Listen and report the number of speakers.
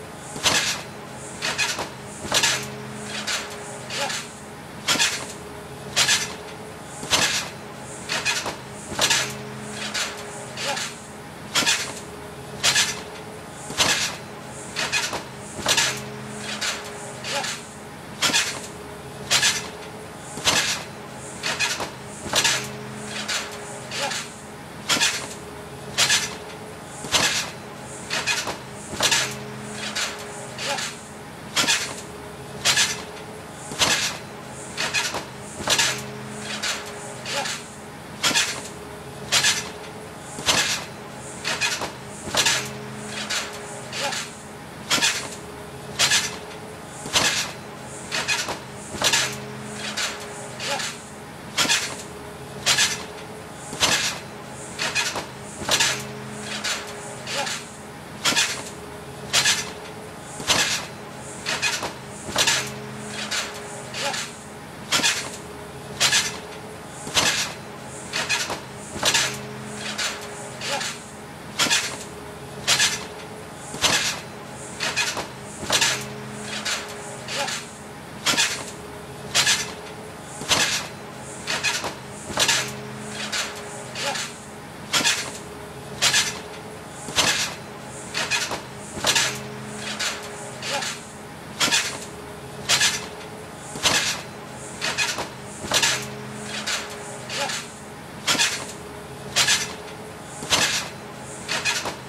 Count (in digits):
0